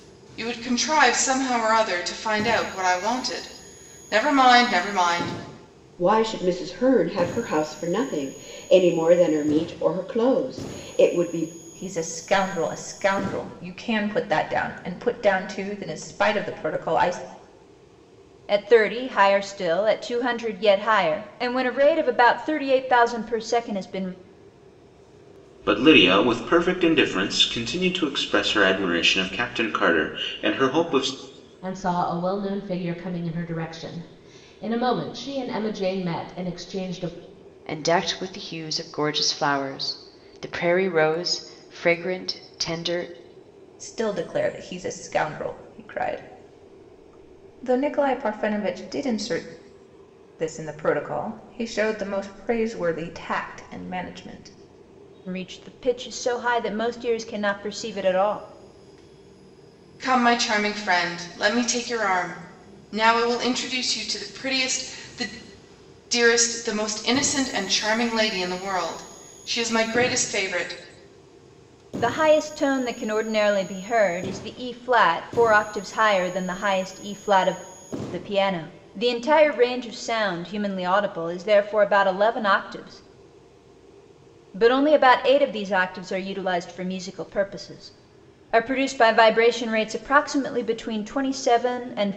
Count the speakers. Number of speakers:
seven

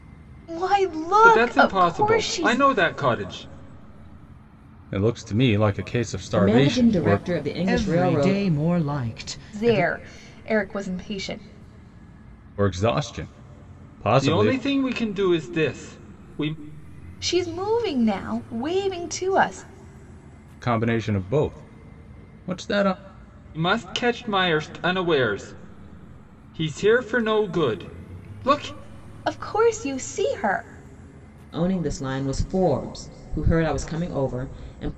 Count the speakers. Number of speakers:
five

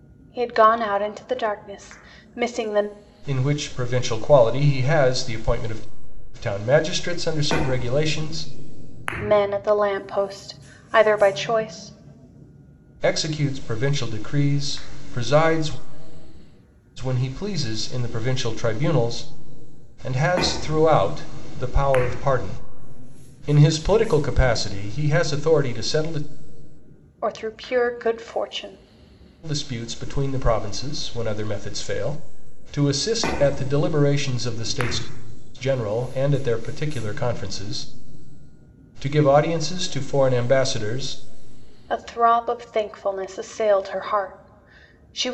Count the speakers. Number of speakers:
two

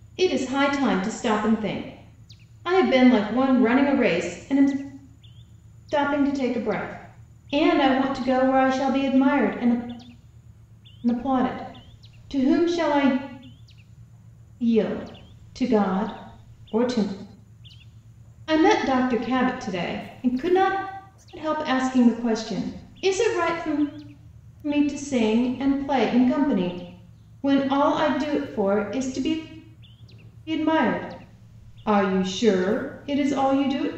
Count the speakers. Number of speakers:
one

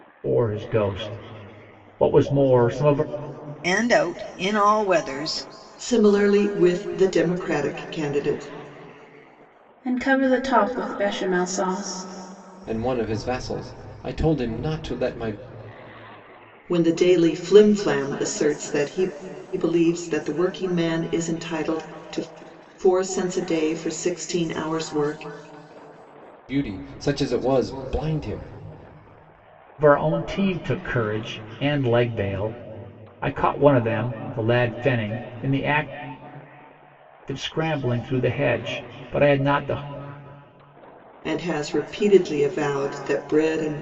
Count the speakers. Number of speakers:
five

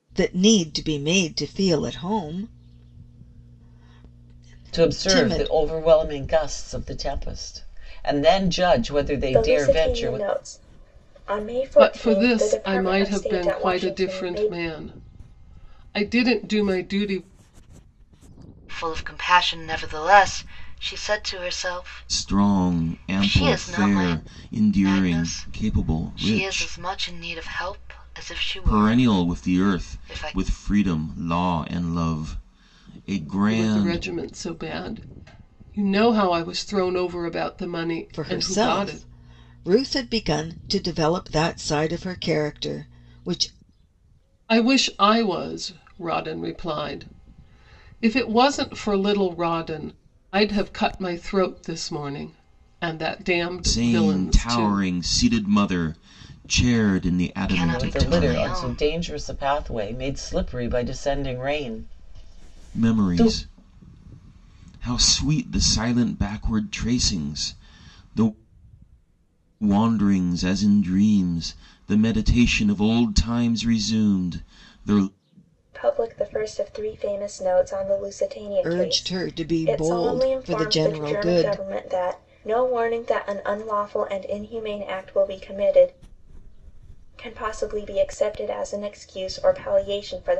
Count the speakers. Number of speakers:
six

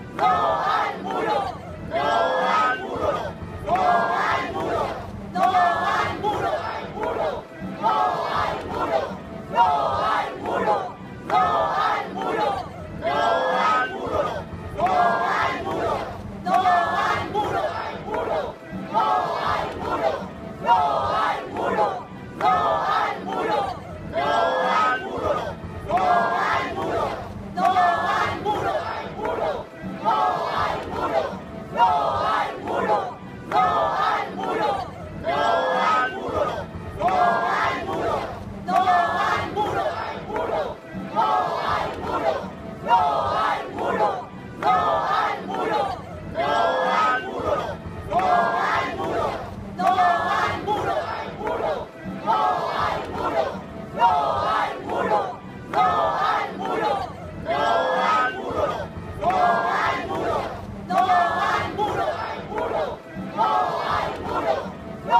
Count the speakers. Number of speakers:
zero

